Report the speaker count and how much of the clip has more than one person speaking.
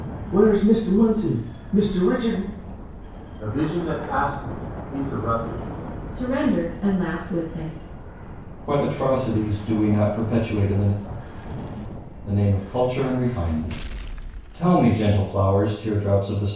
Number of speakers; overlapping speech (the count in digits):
4, no overlap